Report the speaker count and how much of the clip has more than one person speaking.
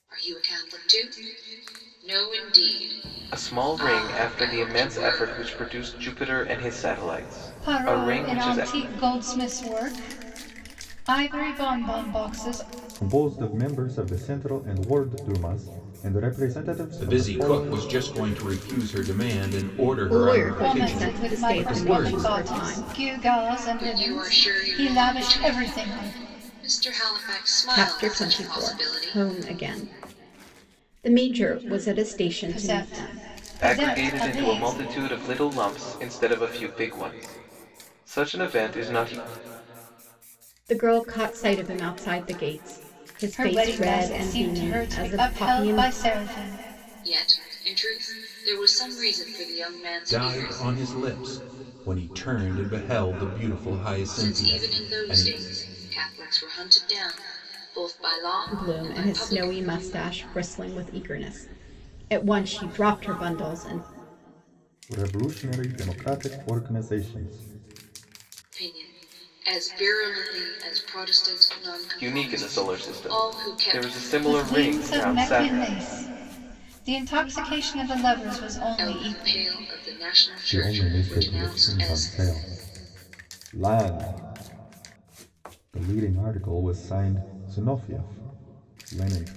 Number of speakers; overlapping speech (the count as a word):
six, about 27%